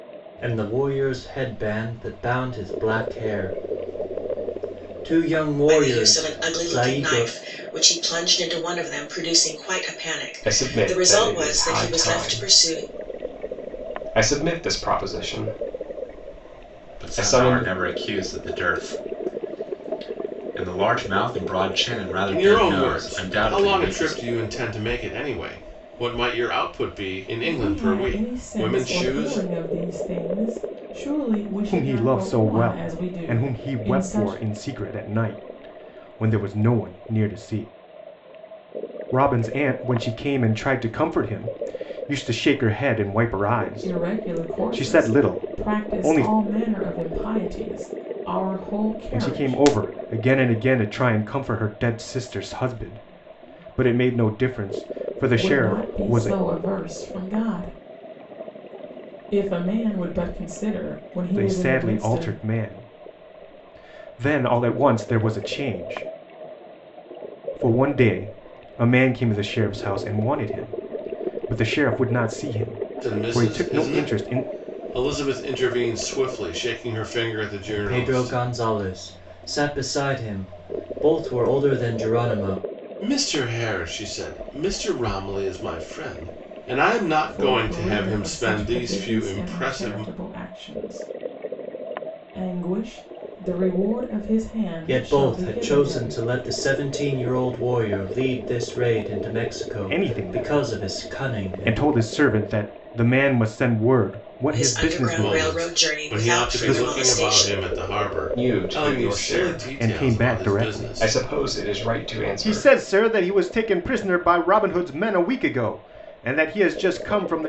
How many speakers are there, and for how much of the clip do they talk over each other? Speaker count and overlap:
7, about 28%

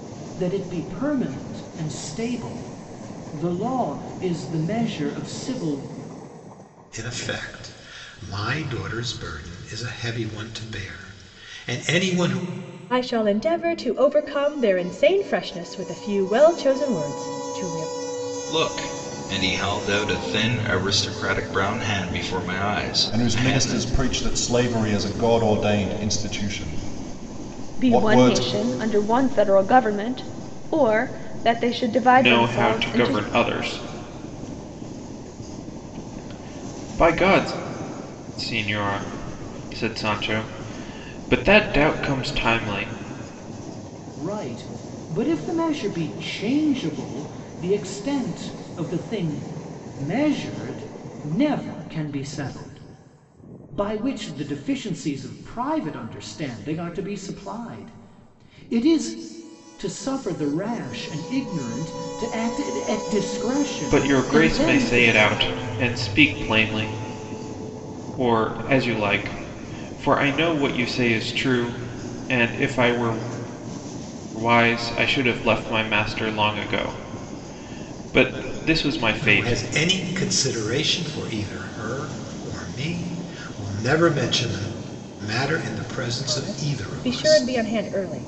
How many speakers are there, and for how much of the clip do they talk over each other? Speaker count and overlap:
7, about 6%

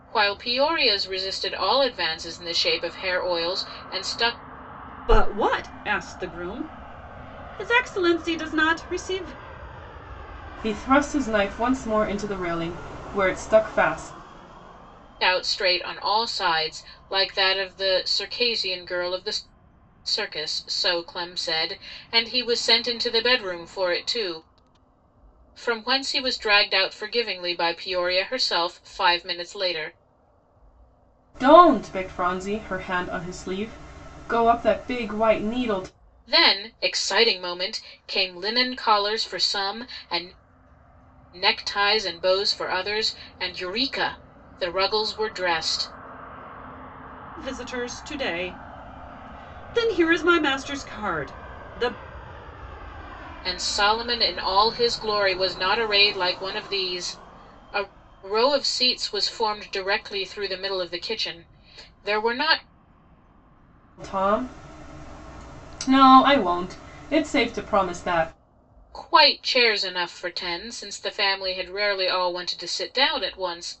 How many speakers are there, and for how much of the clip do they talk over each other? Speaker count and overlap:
3, no overlap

